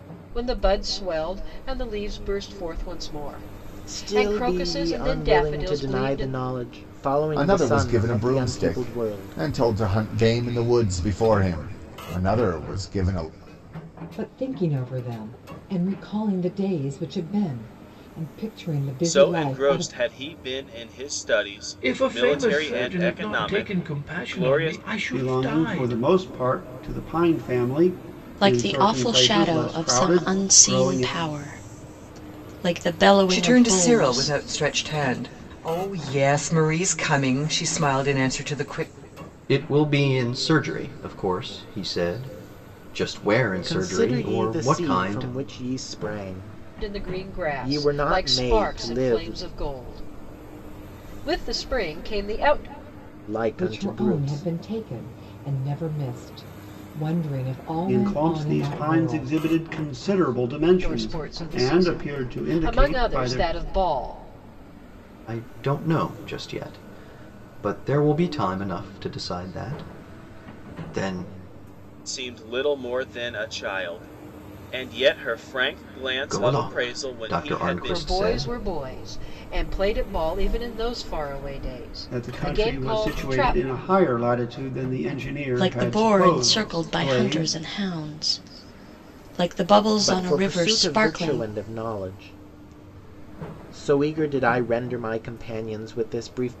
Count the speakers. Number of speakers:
10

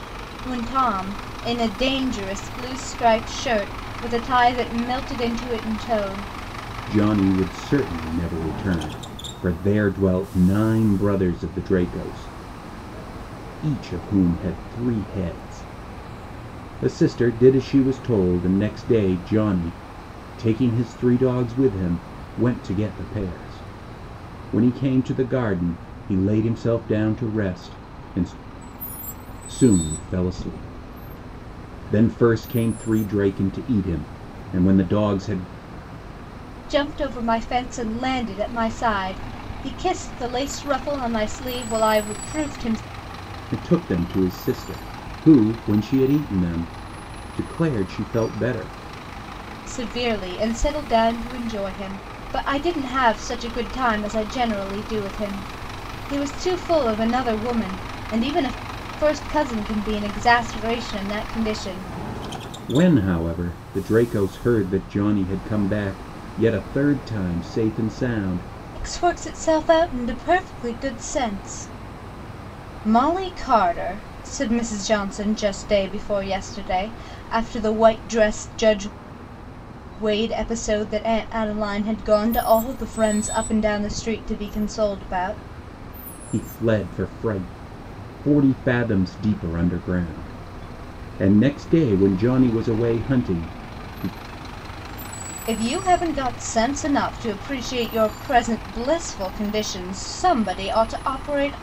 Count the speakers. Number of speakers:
2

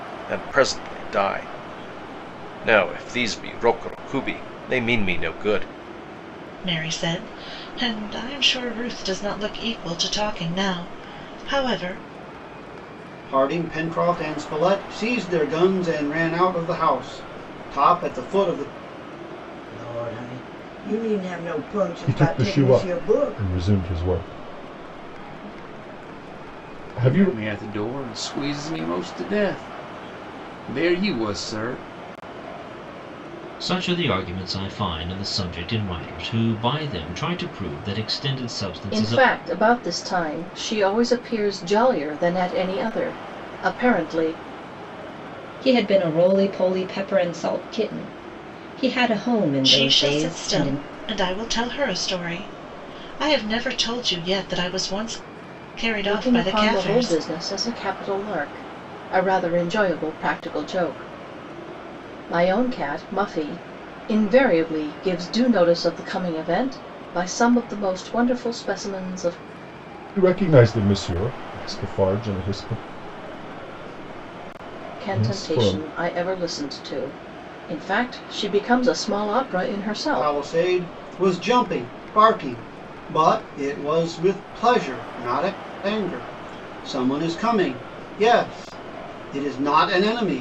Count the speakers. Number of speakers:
9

